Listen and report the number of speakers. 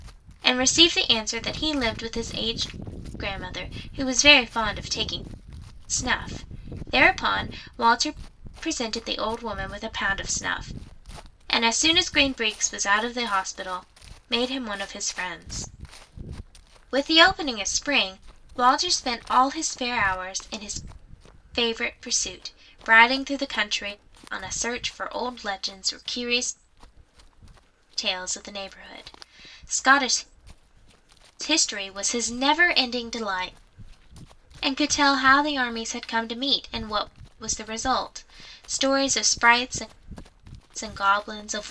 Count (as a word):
one